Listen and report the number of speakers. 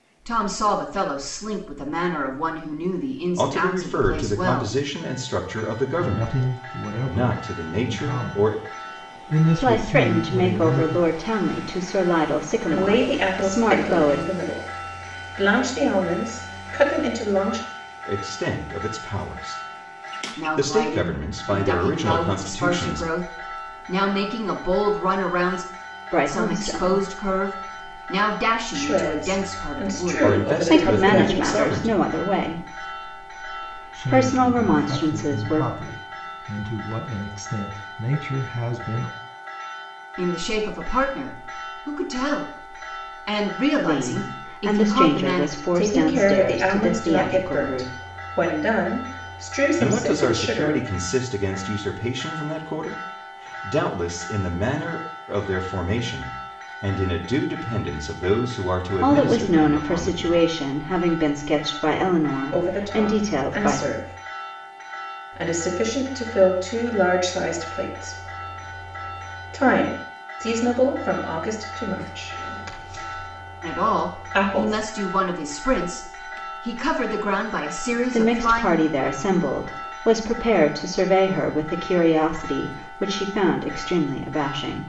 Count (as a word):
five